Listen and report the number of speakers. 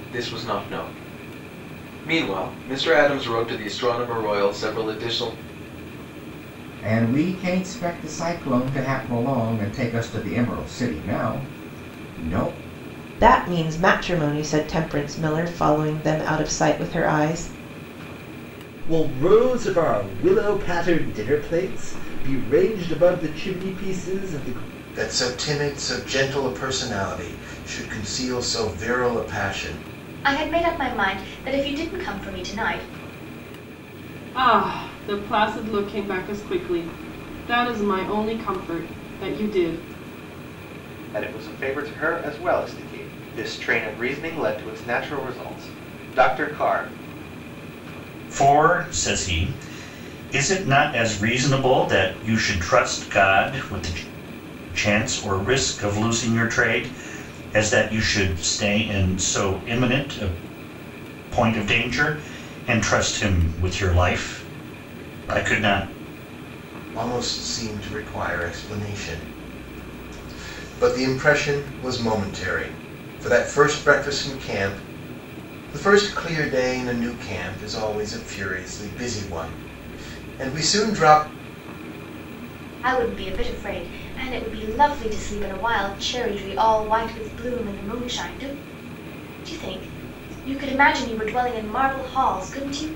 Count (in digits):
9